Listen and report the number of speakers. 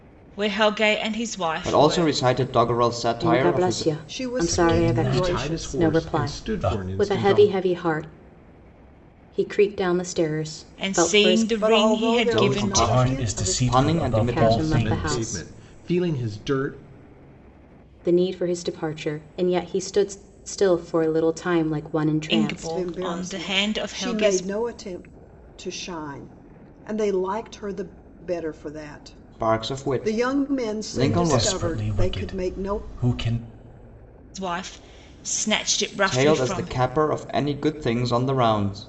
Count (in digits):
6